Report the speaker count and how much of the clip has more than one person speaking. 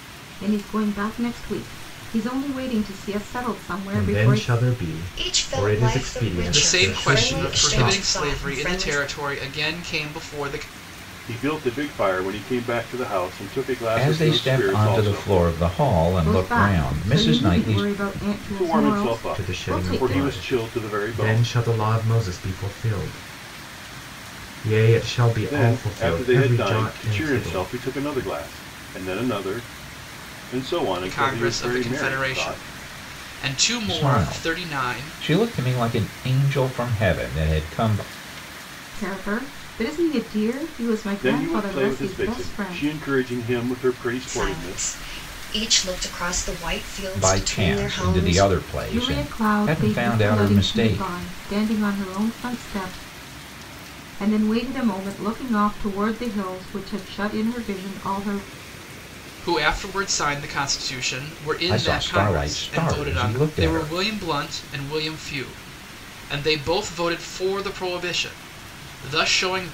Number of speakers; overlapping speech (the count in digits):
6, about 35%